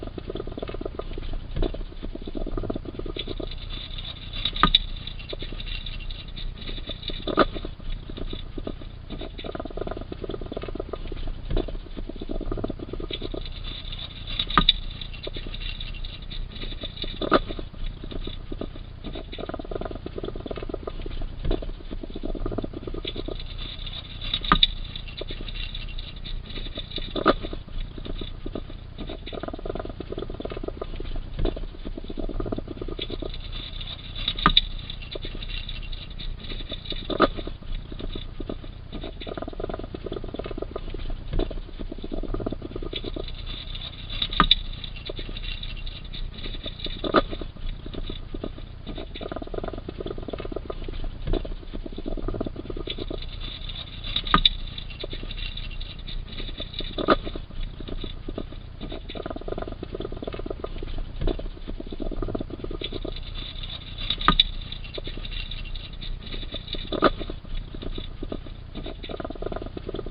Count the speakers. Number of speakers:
zero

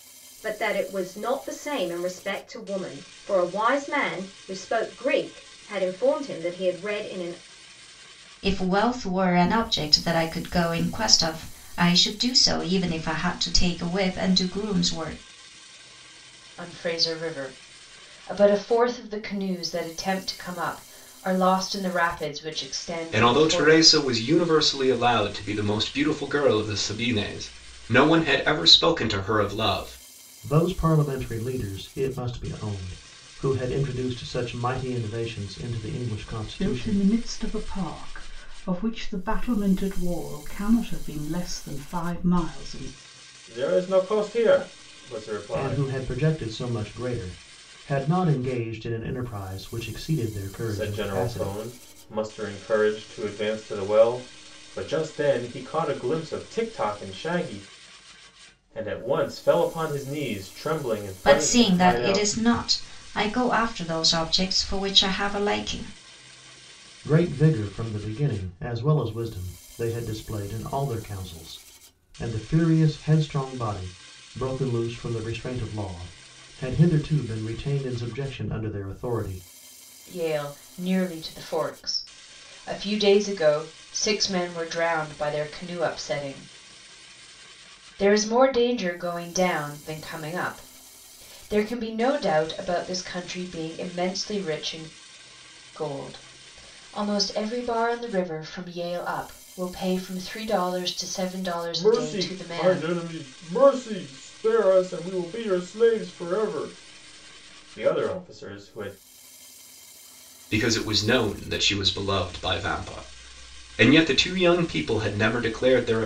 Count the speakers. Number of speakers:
seven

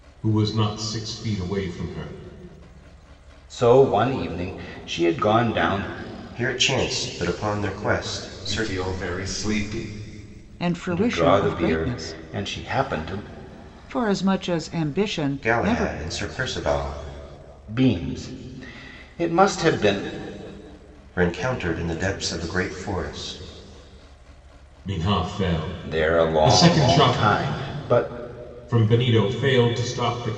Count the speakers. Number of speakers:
five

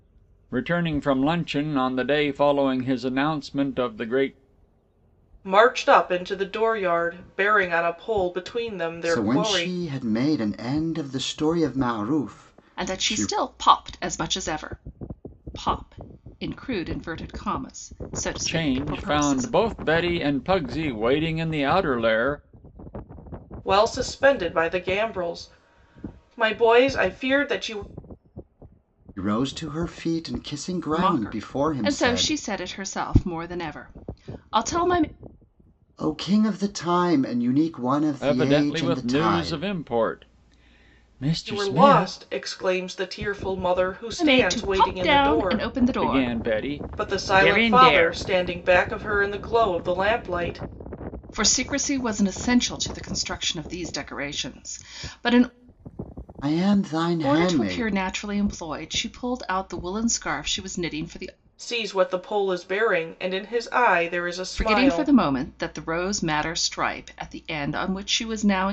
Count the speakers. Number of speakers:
four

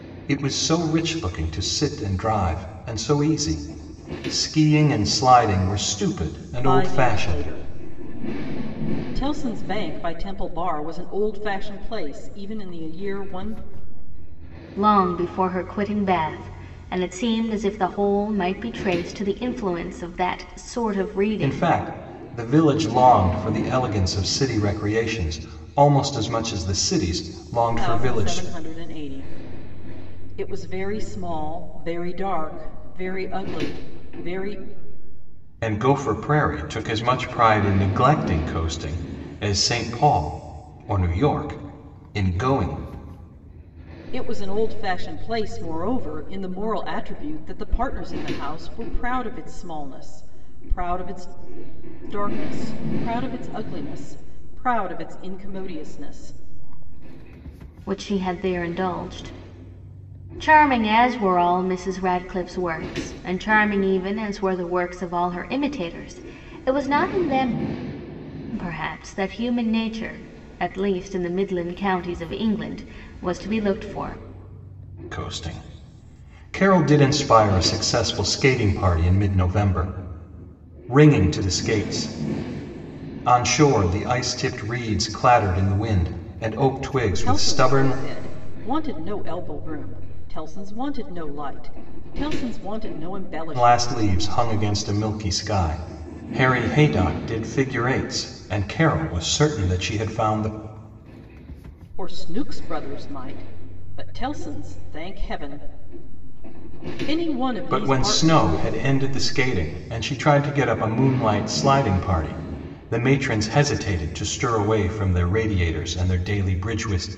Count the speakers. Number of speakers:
three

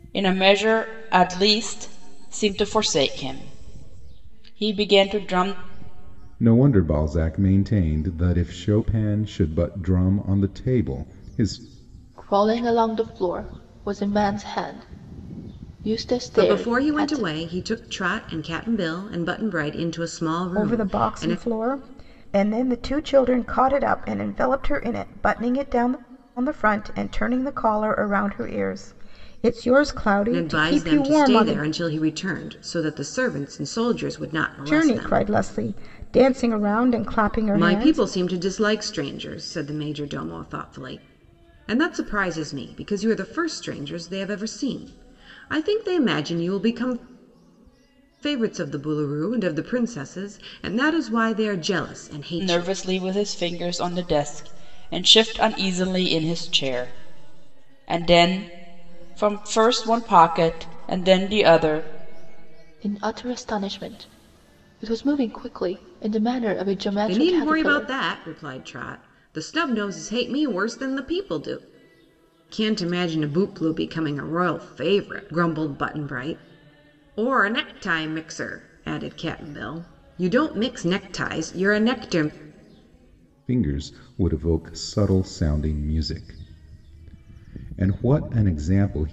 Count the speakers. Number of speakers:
five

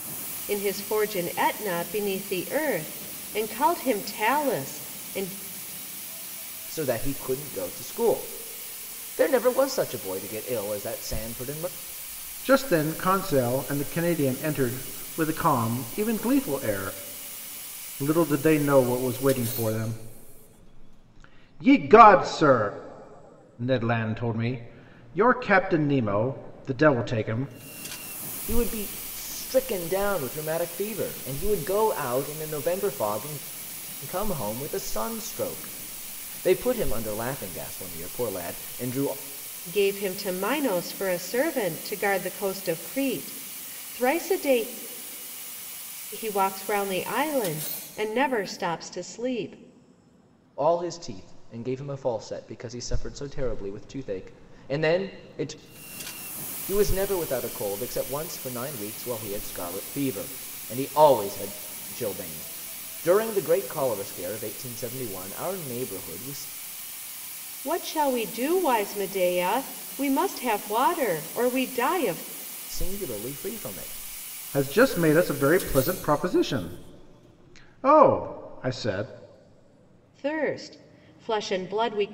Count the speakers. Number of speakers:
three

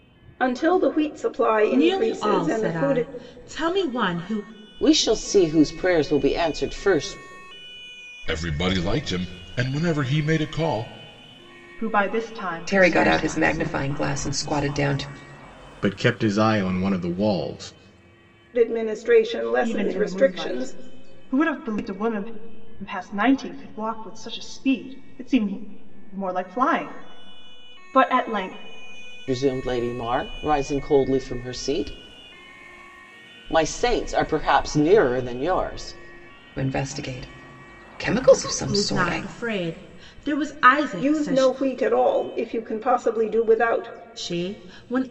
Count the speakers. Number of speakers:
seven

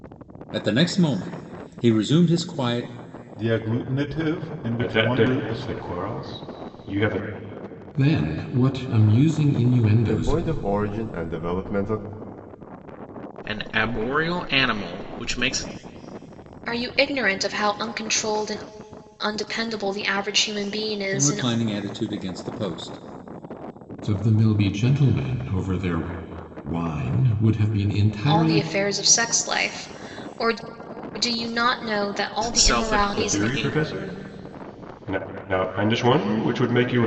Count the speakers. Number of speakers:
seven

